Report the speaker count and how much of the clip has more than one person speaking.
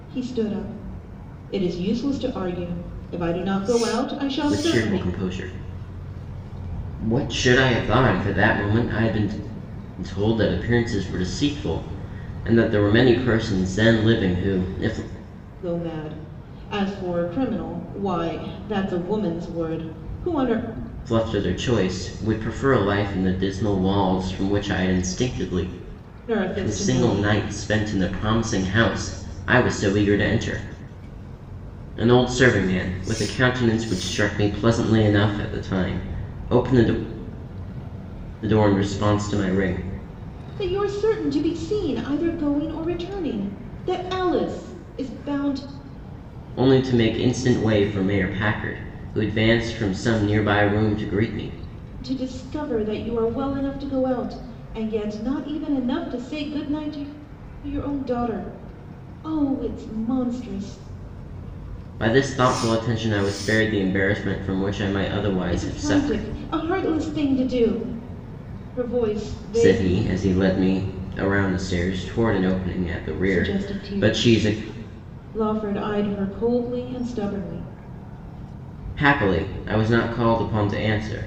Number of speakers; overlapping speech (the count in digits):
2, about 5%